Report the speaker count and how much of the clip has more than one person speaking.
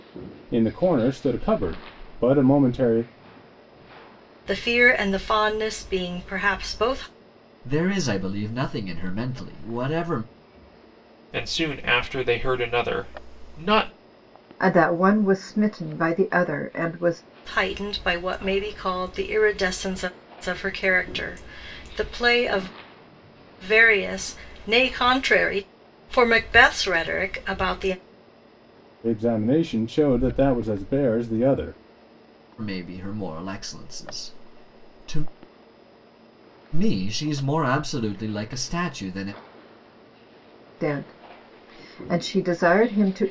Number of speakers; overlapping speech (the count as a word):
five, no overlap